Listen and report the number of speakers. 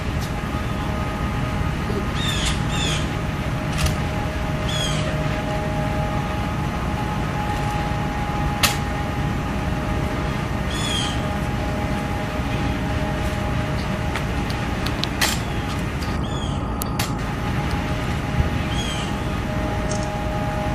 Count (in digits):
0